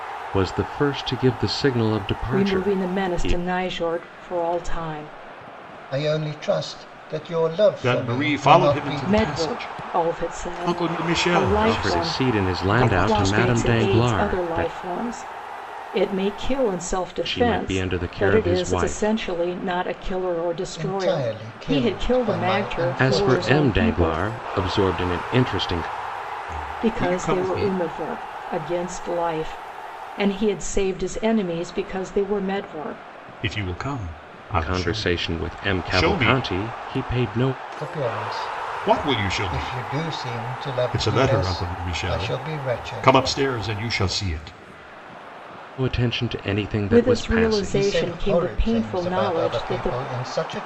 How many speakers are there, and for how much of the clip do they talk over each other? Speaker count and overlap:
4, about 47%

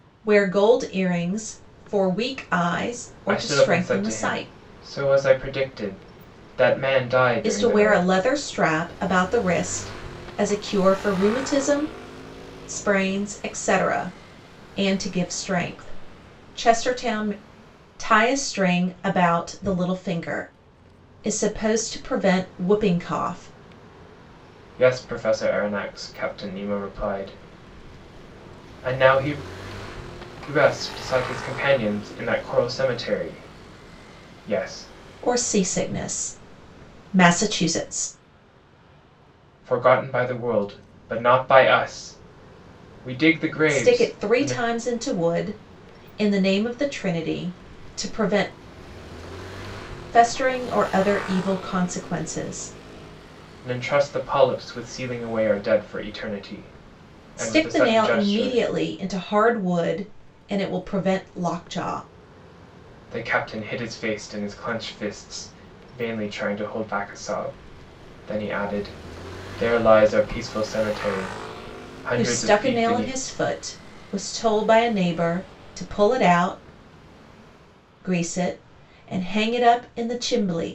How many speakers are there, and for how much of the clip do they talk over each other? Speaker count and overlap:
2, about 7%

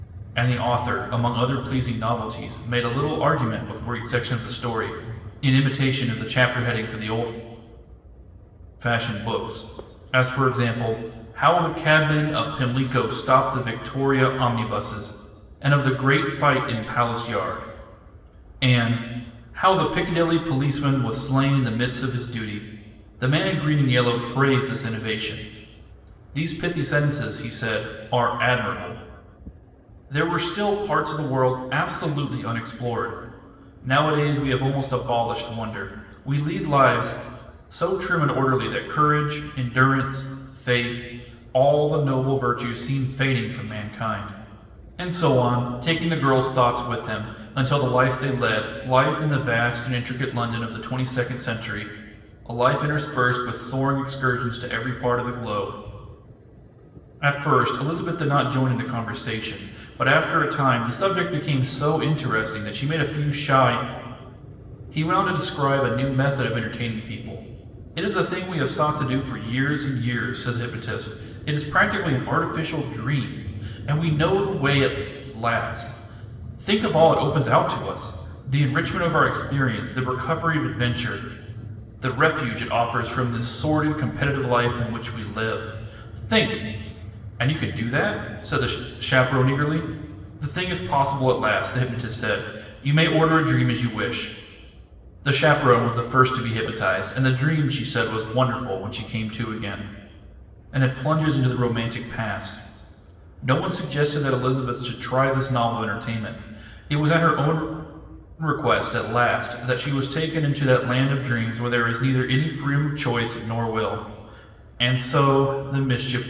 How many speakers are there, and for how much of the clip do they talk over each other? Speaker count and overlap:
1, no overlap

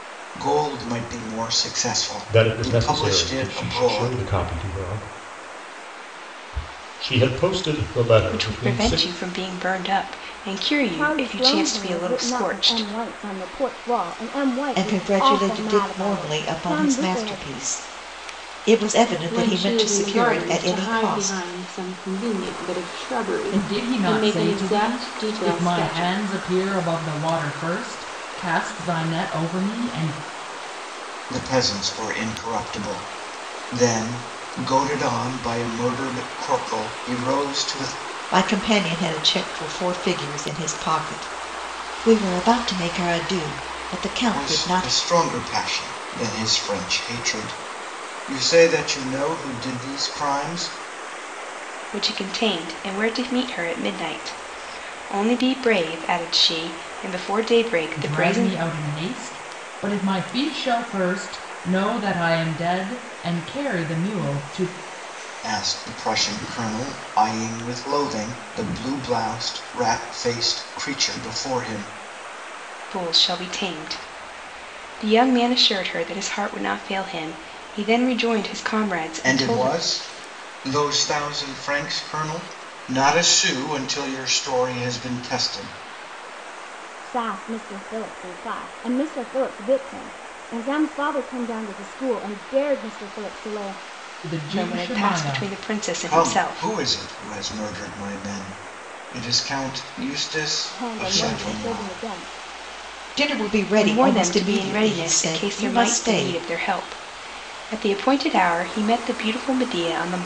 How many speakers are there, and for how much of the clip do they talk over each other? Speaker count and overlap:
7, about 18%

